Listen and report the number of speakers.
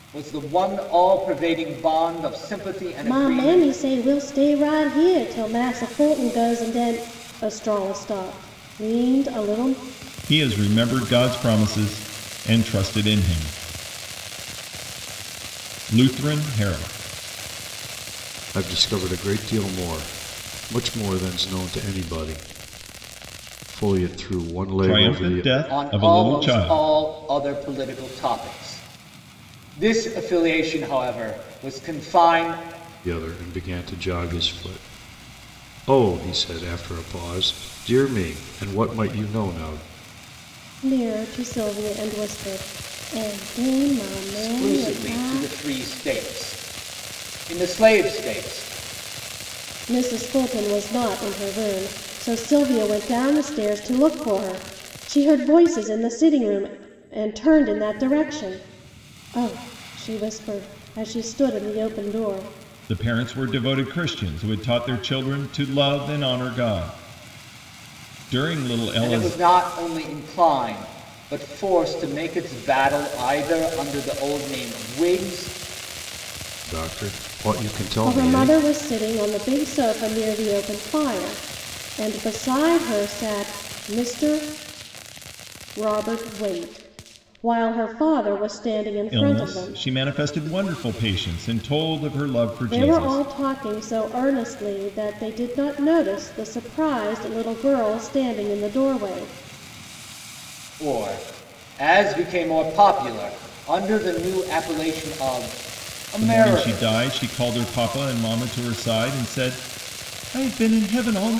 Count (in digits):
4